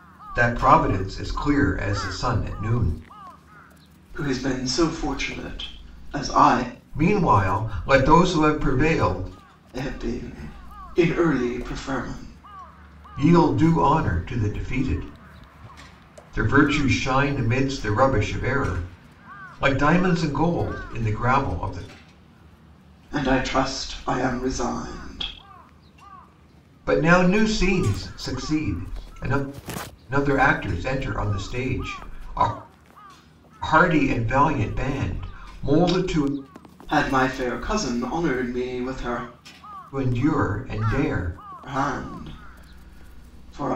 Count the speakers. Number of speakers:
2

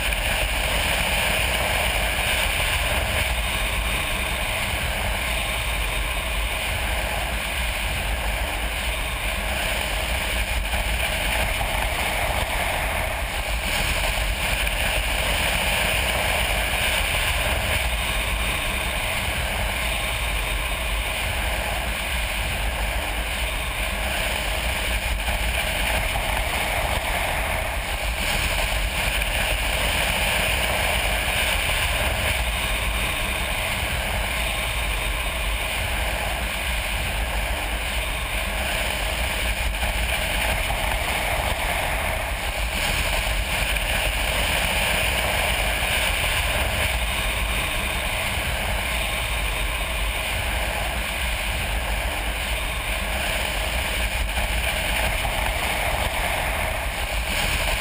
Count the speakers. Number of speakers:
0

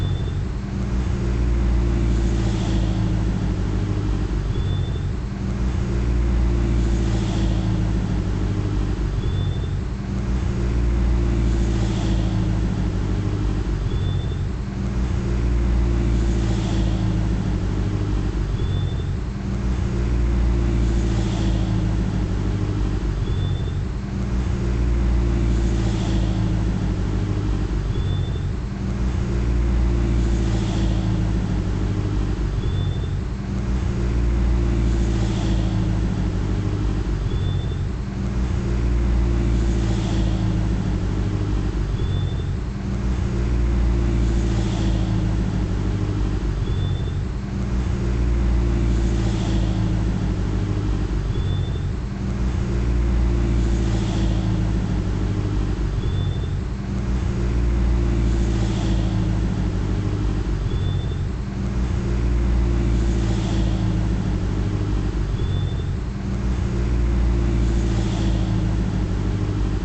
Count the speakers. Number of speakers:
0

